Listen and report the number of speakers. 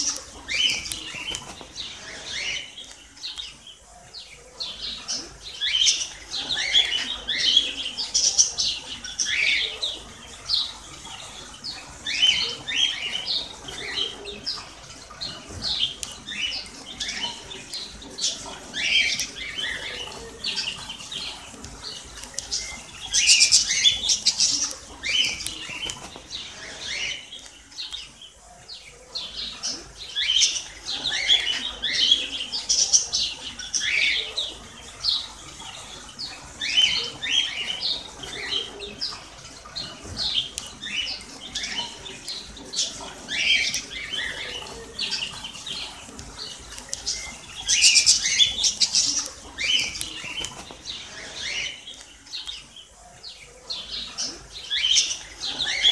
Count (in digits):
0